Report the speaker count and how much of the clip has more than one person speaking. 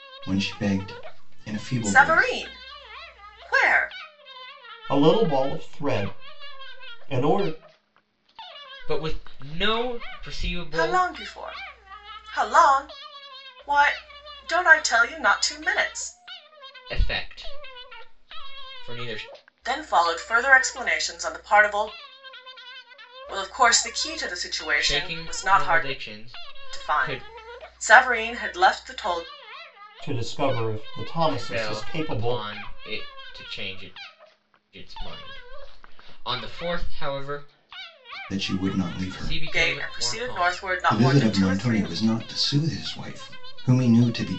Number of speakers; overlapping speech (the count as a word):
four, about 15%